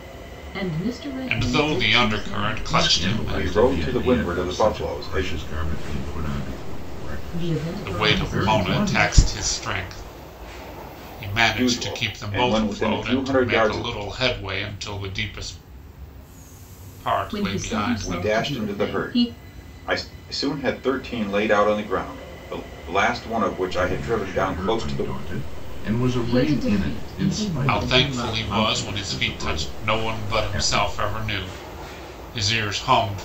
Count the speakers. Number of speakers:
five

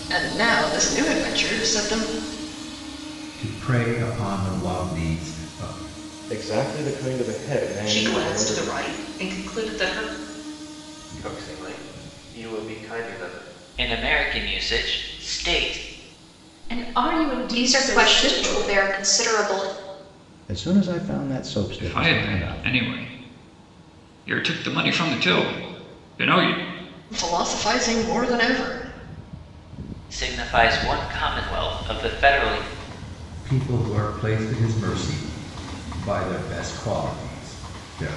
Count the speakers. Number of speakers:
ten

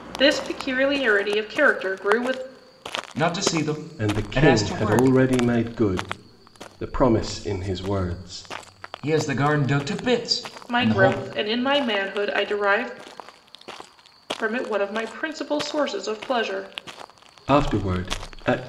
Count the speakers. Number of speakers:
three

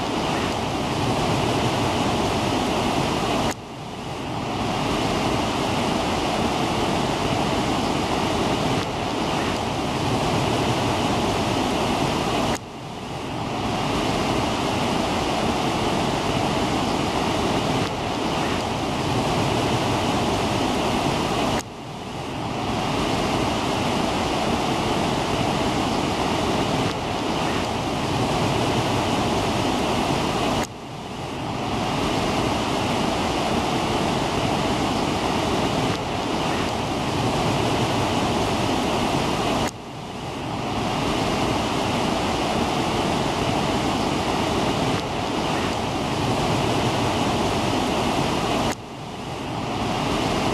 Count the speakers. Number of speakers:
zero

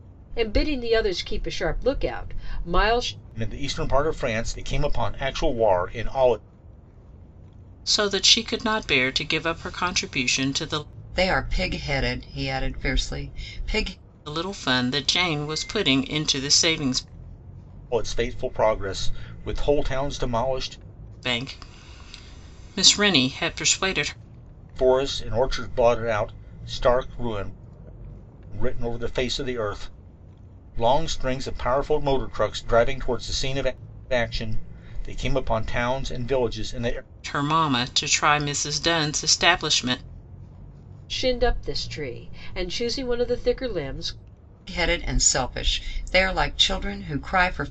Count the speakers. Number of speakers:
four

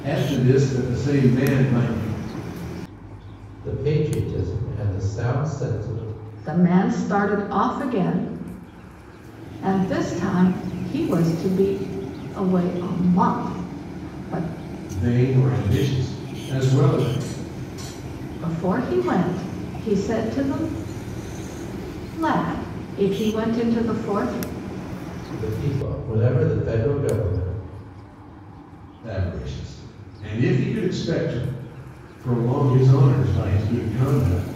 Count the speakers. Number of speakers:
three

